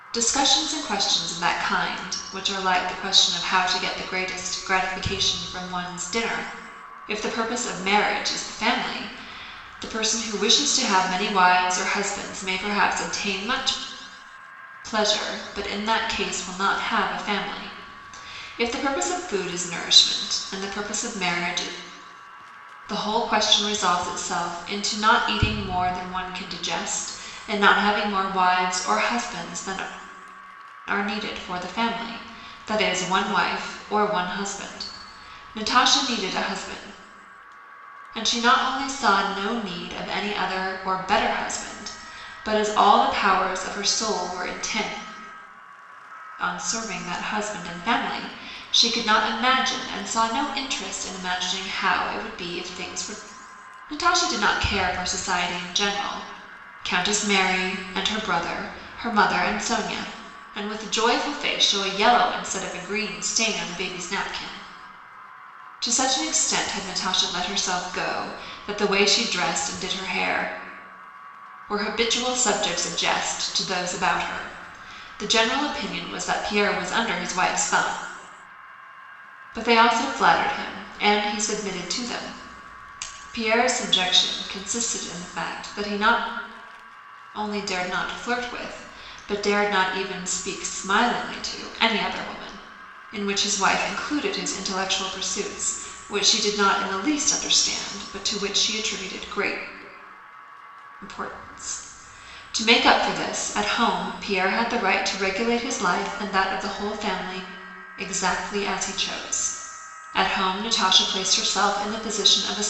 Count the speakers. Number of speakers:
one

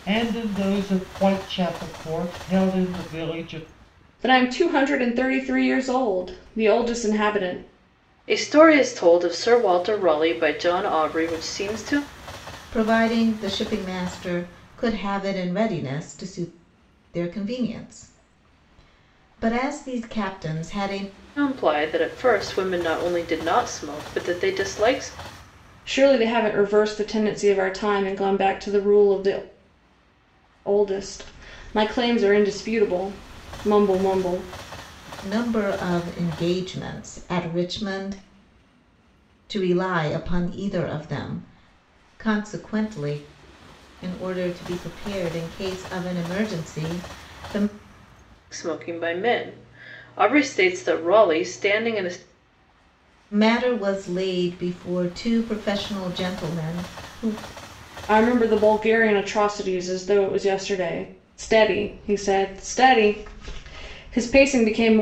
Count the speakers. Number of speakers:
four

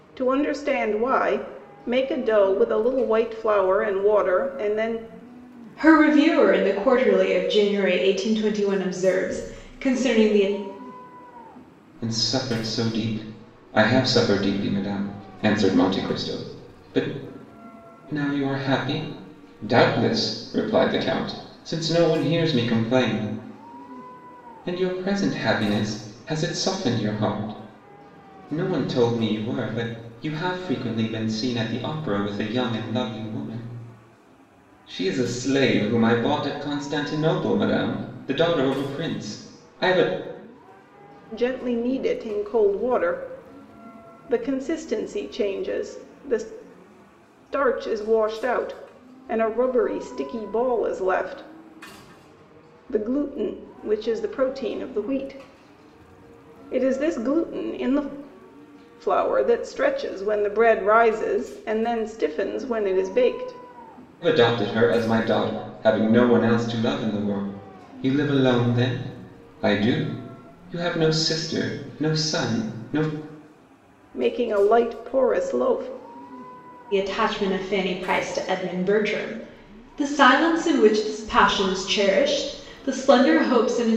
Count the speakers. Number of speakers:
three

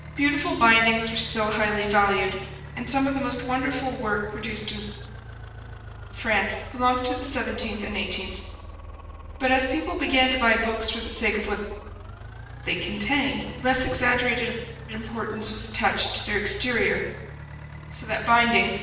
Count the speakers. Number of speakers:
one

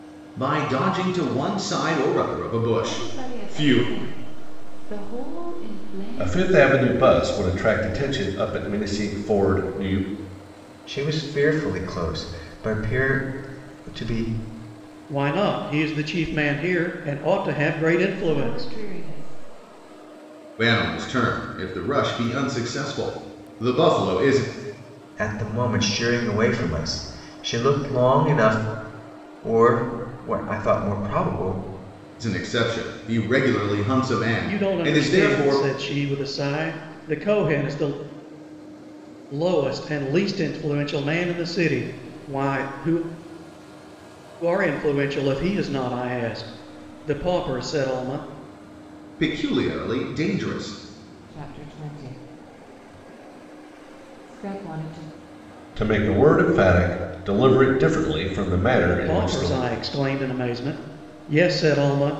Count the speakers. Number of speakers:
five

